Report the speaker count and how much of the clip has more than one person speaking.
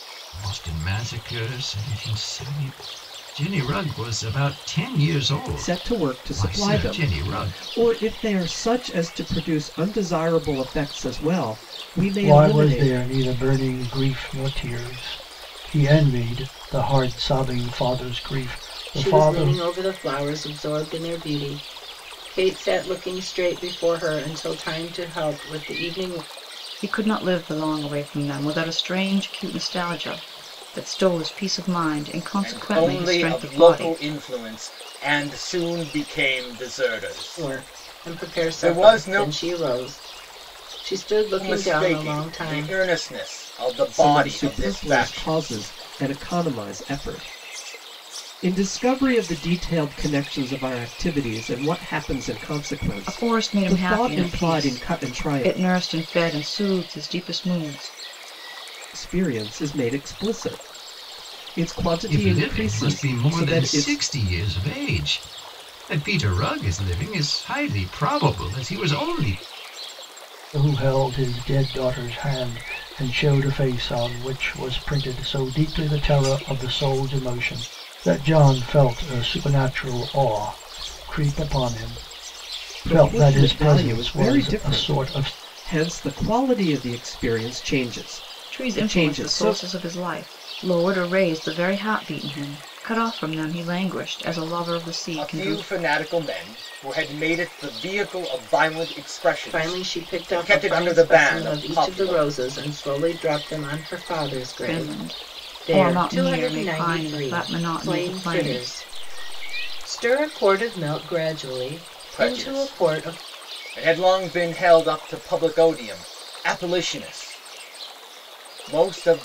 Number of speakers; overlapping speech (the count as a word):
six, about 22%